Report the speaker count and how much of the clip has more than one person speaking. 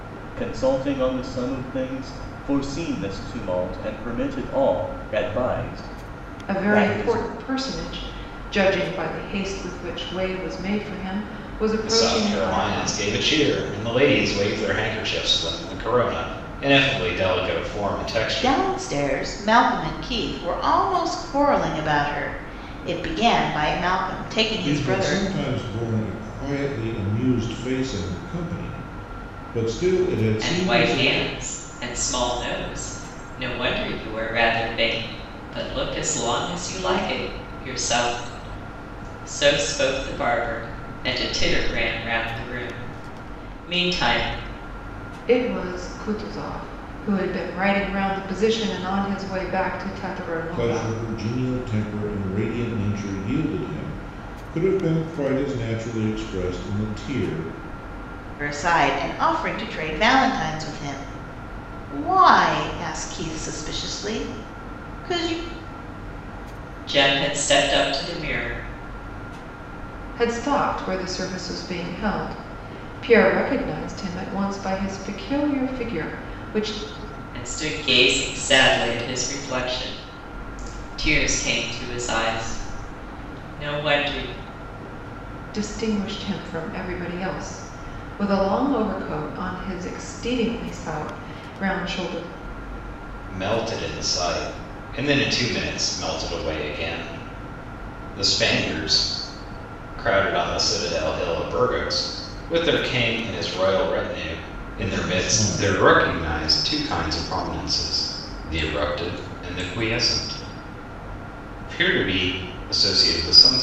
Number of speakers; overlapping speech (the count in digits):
6, about 5%